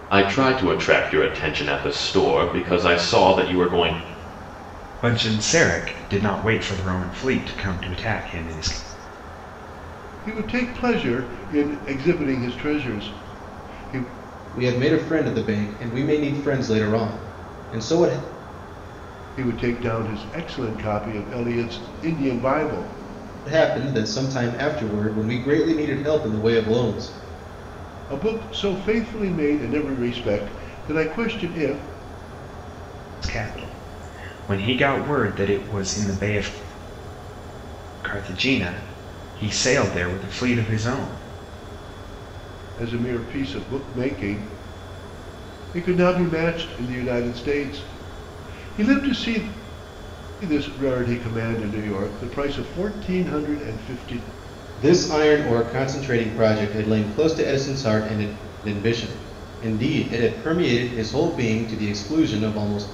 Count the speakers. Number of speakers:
4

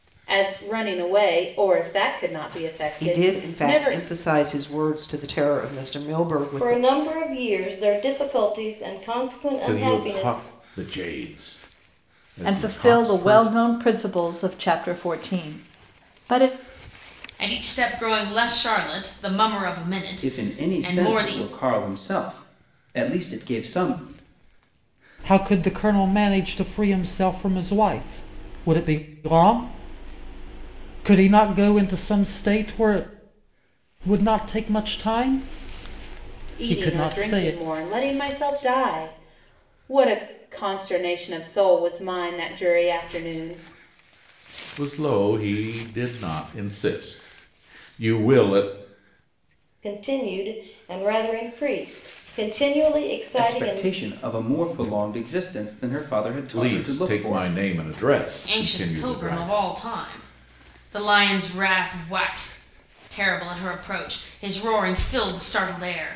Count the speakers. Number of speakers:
8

